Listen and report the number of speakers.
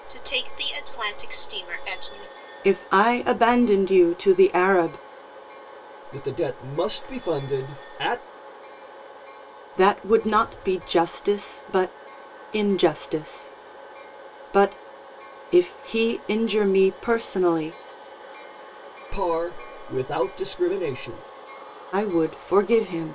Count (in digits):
3